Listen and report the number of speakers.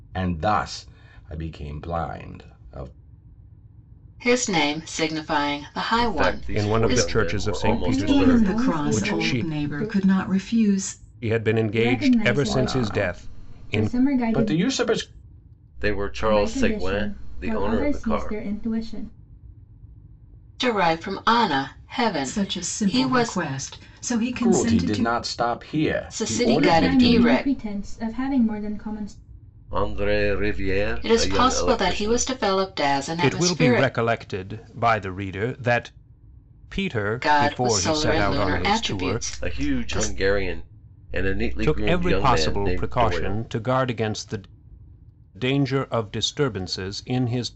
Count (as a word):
six